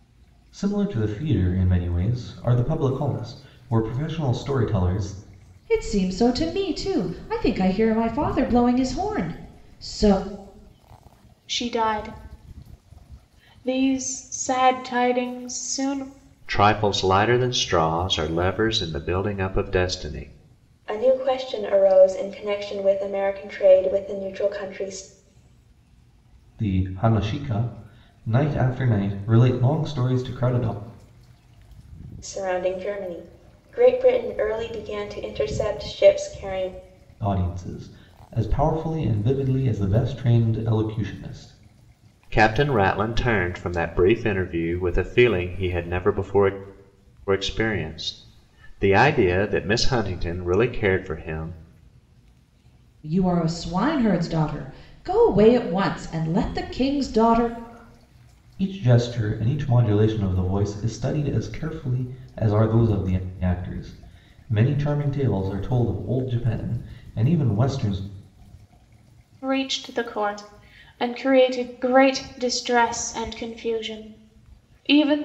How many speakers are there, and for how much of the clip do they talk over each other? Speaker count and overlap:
5, no overlap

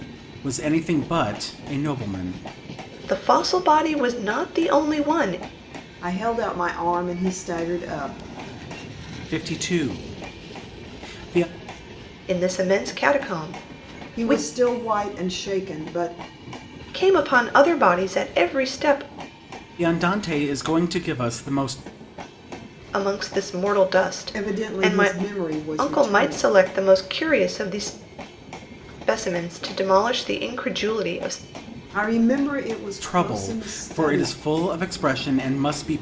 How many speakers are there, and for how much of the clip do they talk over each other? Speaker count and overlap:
3, about 9%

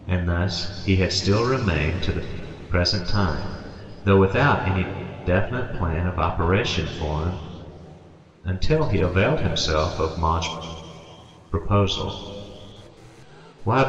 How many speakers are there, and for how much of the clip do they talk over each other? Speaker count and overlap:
1, no overlap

